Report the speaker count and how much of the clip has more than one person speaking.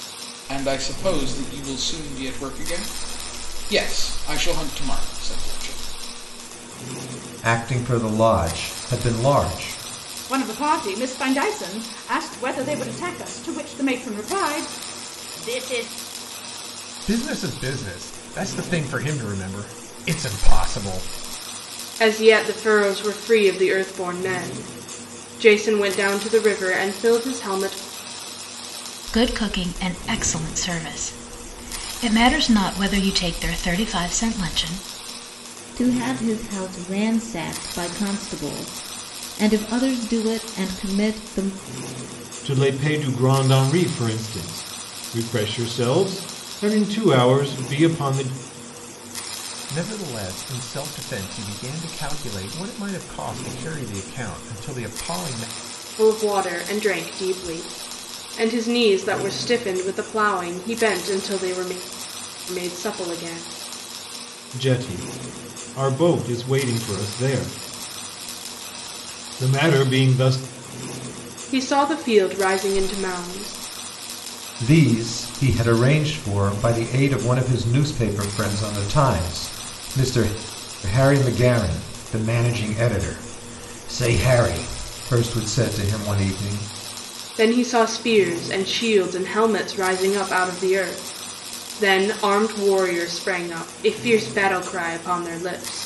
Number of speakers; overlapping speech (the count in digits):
8, no overlap